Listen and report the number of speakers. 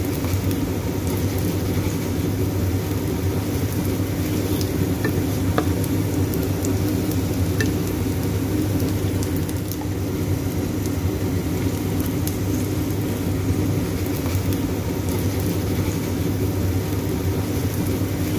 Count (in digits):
0